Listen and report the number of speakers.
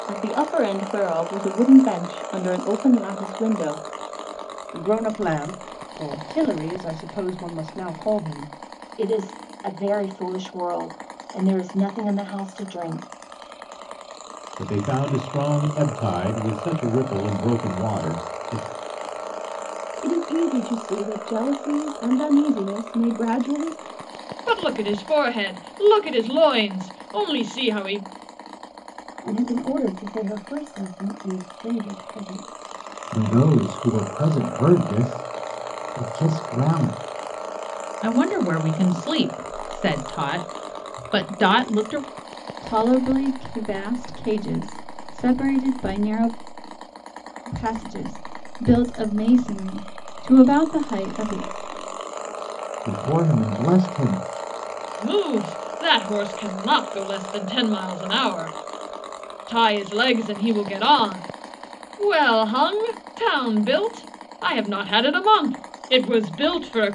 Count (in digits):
10